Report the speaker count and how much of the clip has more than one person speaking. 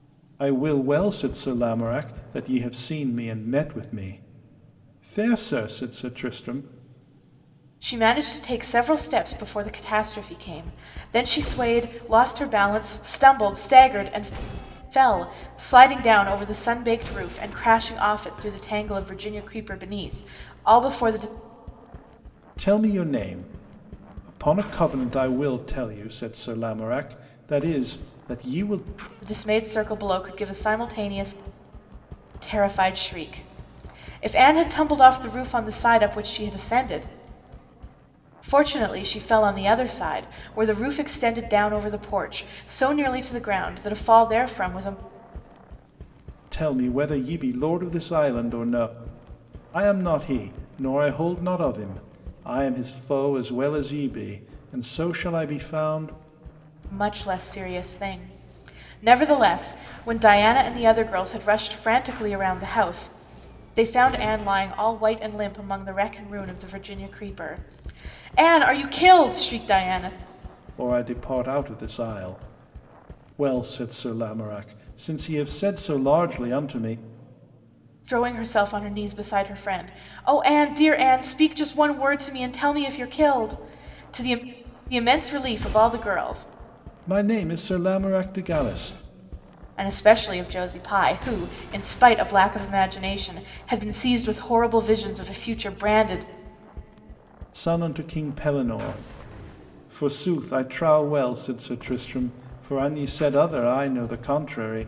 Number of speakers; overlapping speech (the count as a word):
two, no overlap